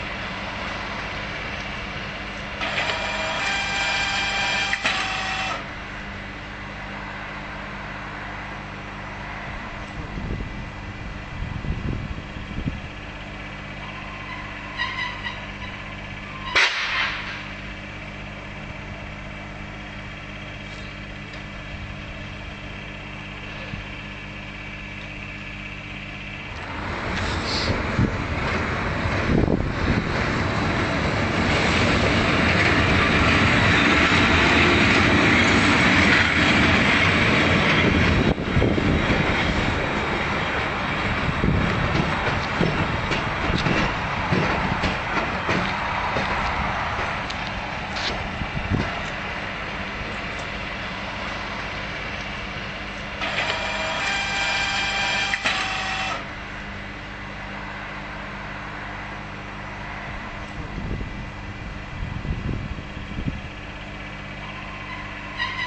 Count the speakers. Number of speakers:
0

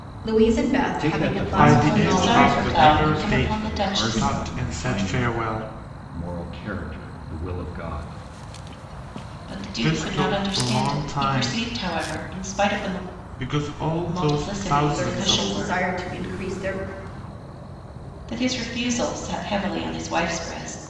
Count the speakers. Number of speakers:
4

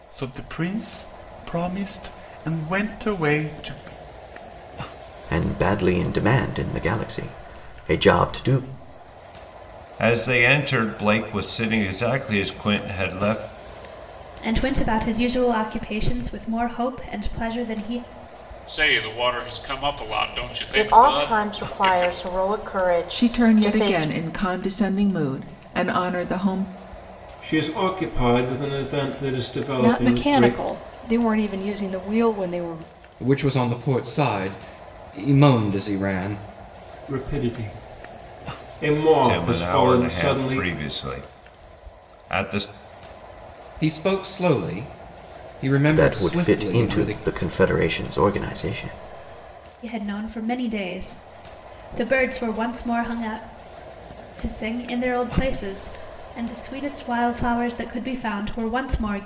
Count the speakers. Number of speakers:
10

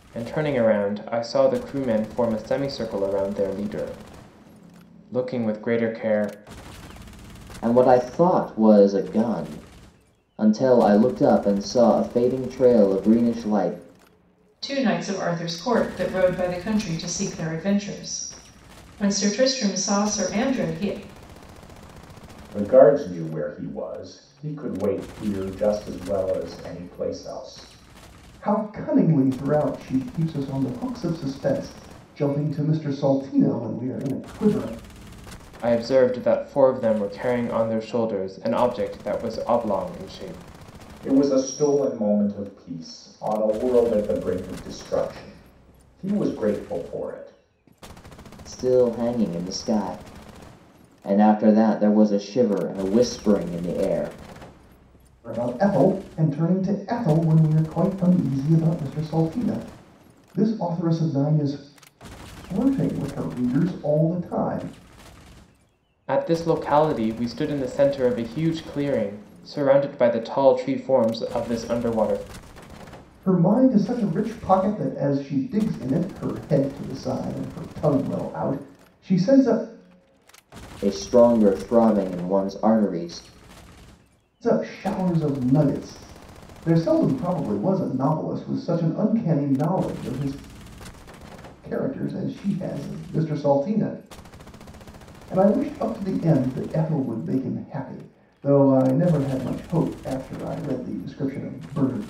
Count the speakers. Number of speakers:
5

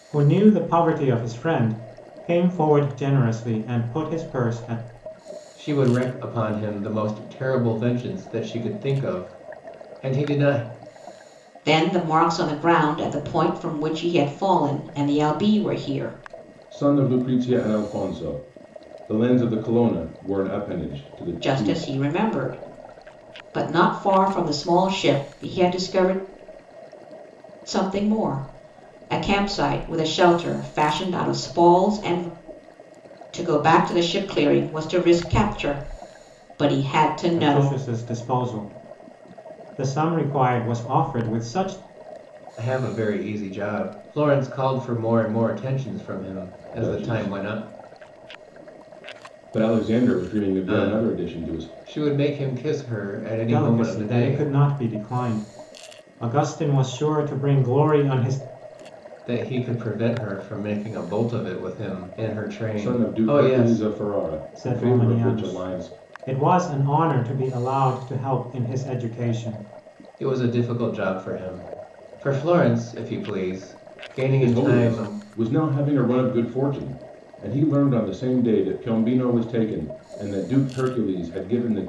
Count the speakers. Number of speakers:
4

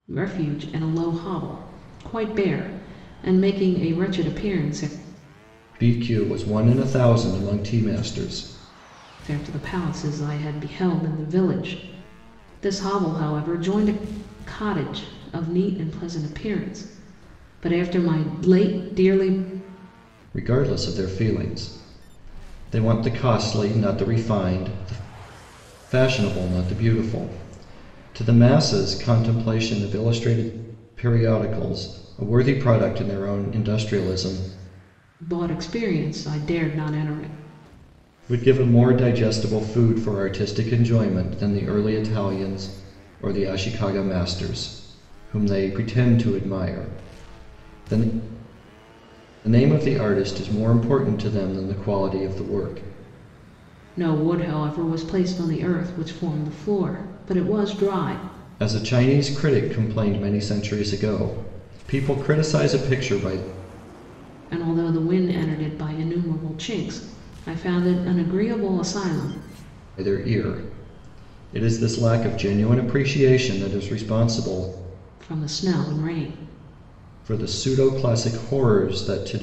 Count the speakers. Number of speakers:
2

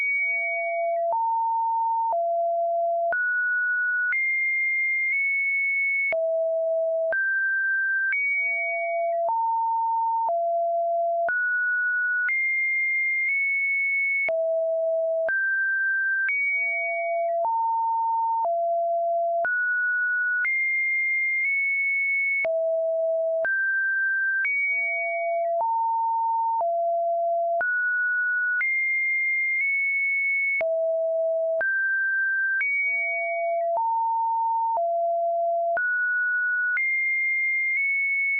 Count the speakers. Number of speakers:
0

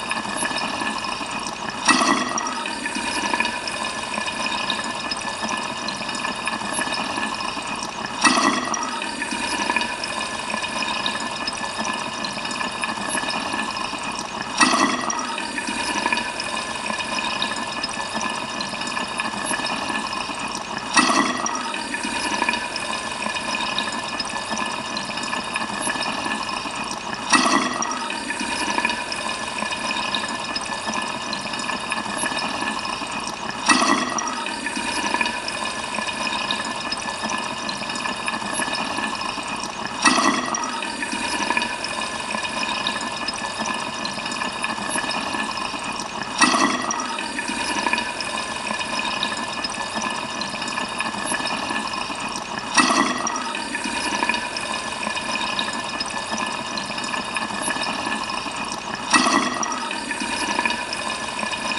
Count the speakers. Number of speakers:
0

